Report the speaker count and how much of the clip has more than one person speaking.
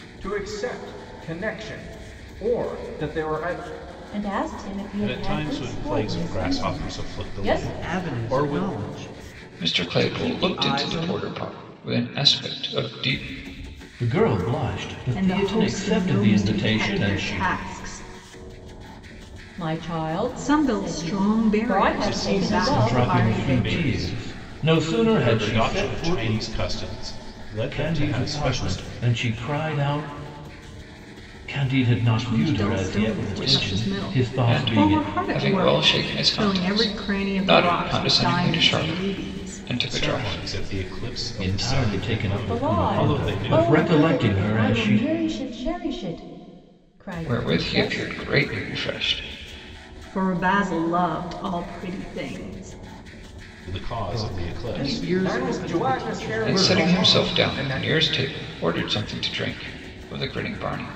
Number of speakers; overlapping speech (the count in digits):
7, about 50%